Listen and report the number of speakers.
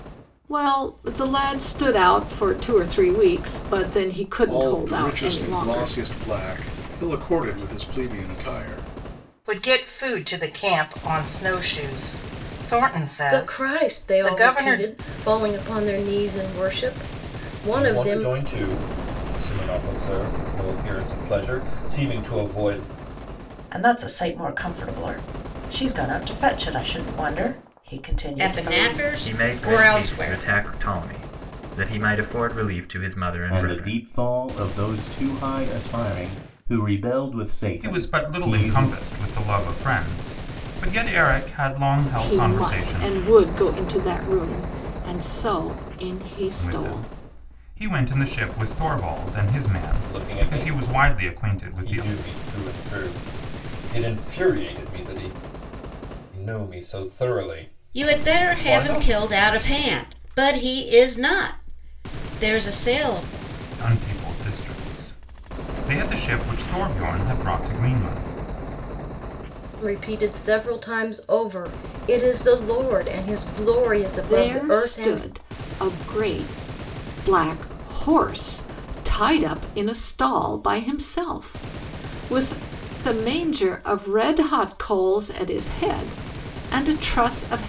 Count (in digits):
10